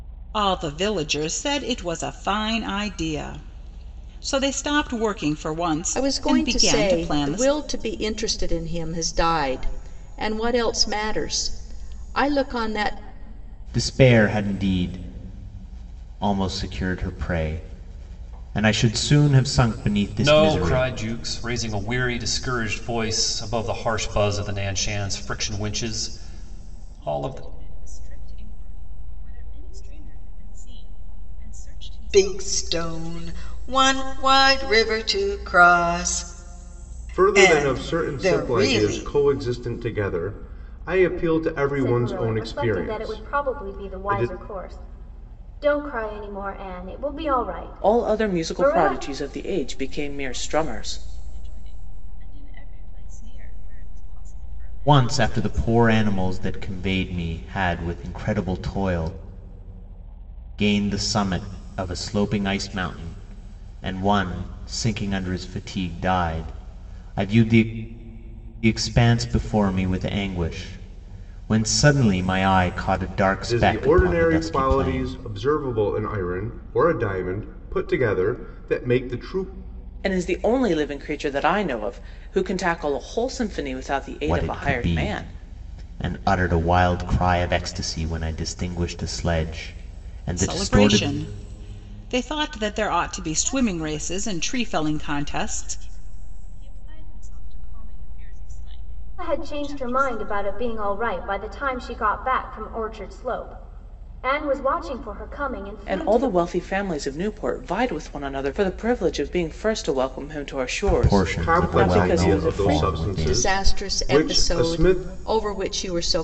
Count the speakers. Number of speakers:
nine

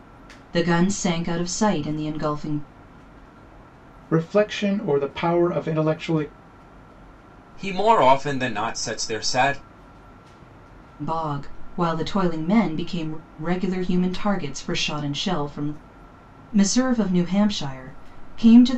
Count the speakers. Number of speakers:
three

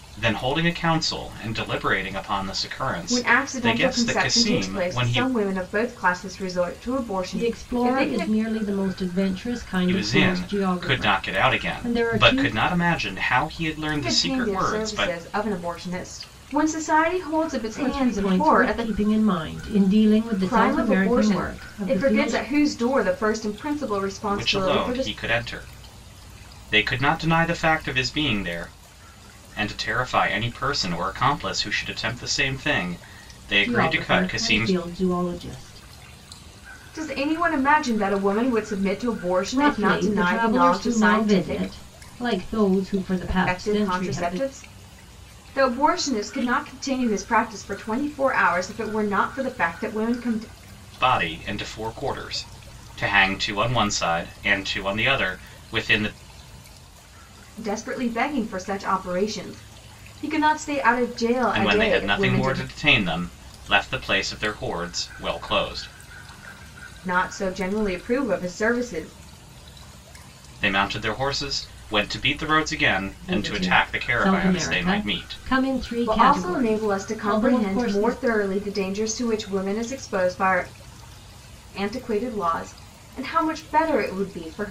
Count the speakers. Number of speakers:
three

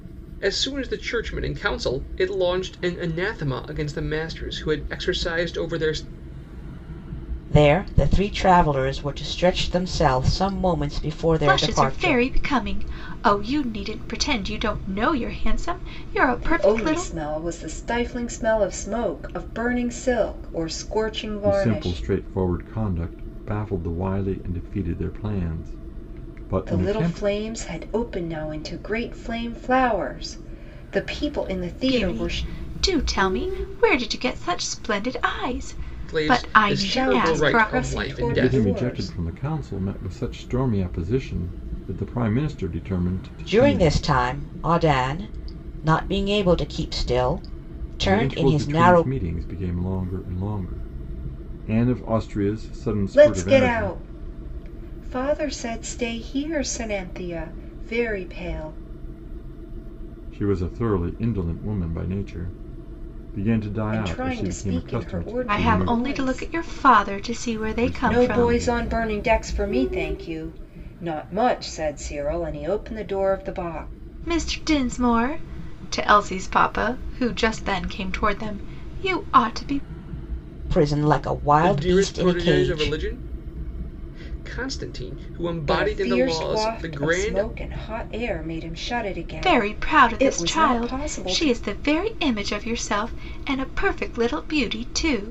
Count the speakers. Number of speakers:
five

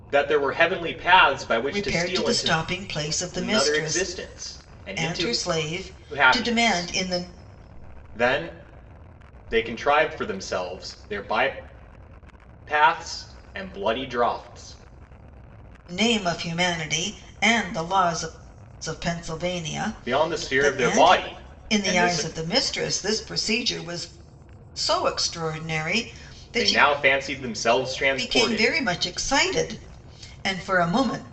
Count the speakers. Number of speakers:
two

